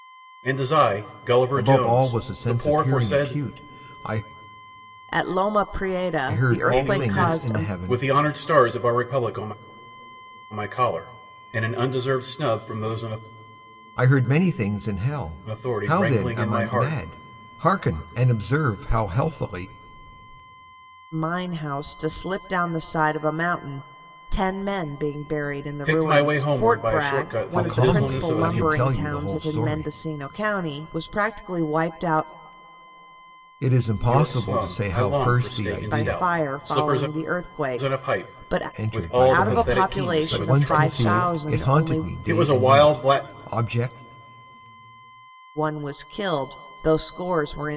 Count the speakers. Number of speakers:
three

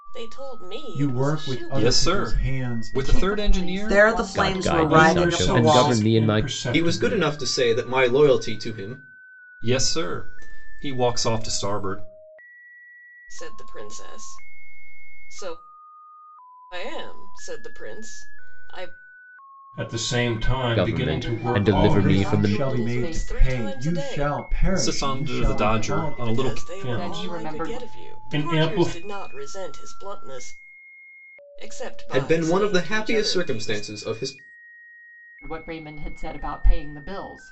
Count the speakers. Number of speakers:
eight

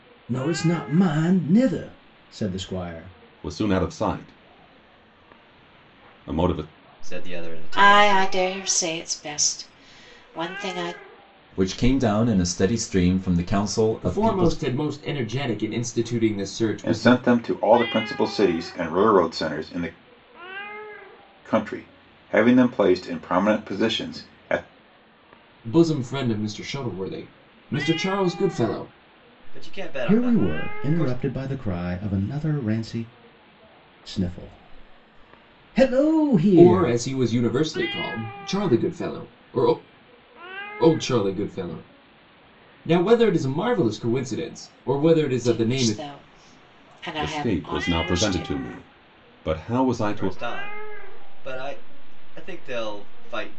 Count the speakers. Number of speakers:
seven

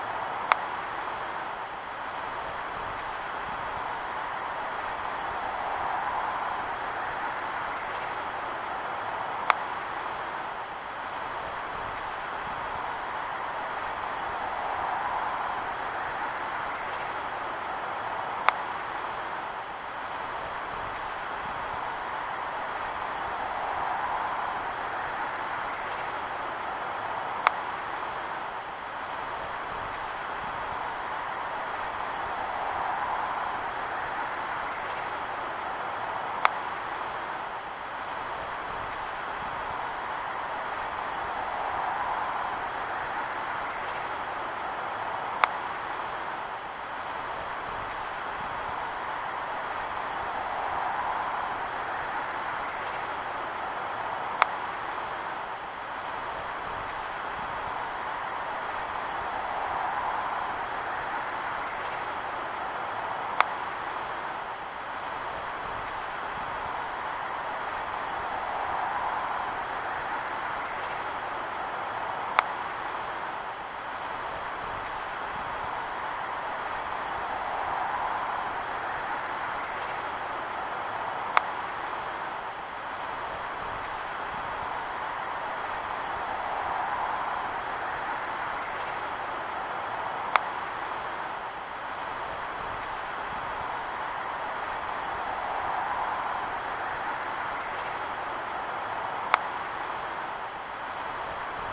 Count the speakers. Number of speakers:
zero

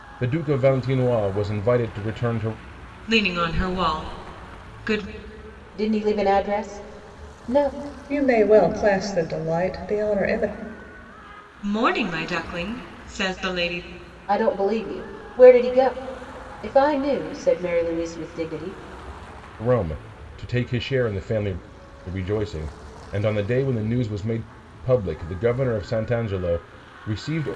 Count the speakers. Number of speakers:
four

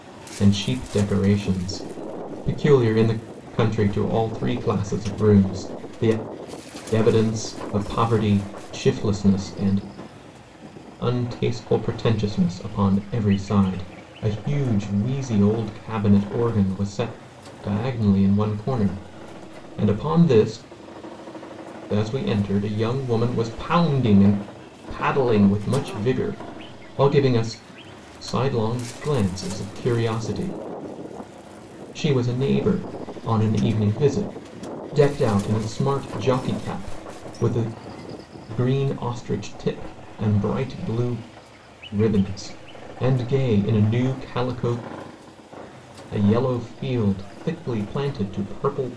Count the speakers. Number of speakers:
one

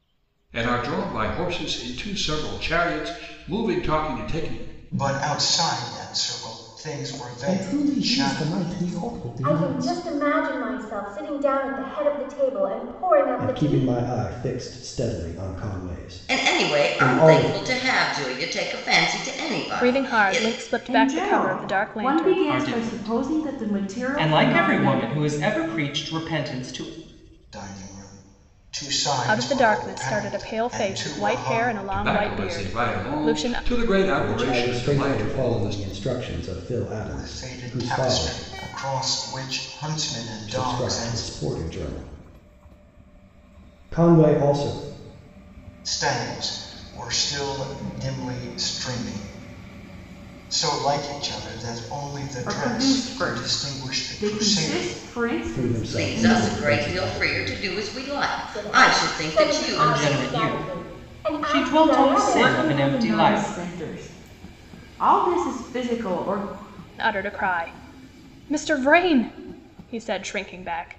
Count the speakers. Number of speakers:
nine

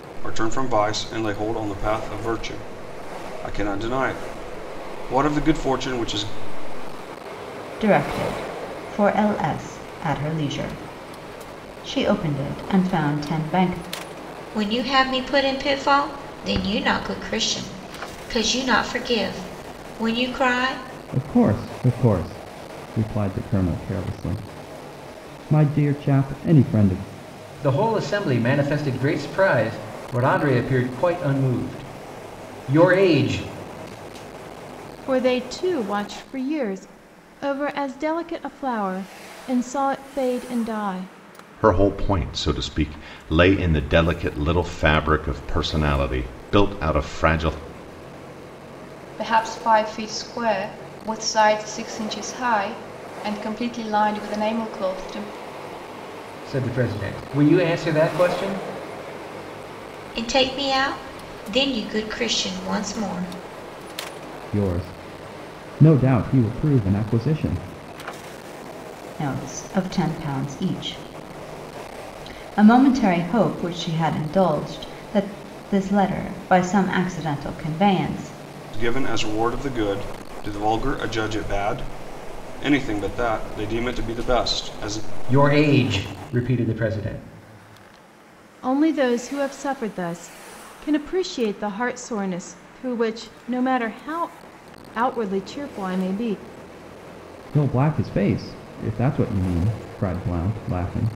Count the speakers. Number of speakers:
eight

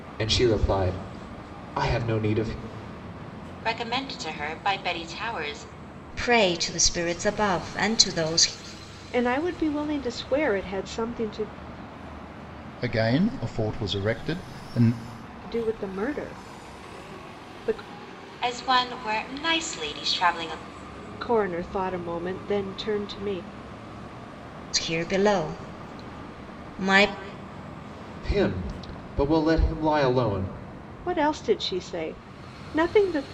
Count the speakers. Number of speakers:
five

